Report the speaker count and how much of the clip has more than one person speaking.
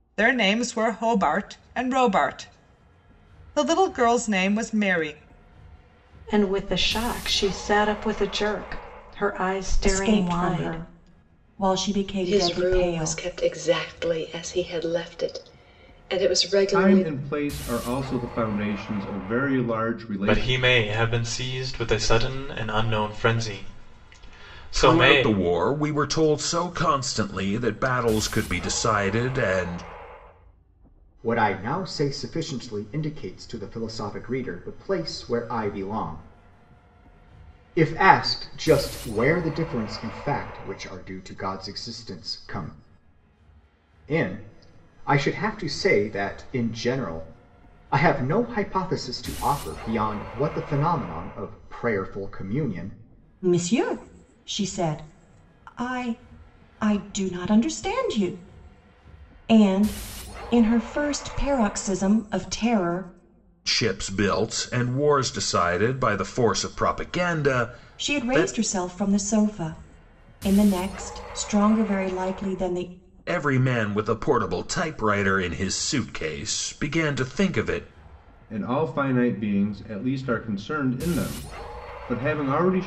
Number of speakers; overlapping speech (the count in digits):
8, about 5%